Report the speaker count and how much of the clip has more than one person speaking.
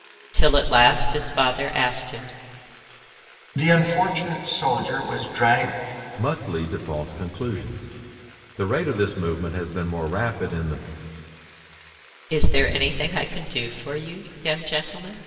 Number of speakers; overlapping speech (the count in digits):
3, no overlap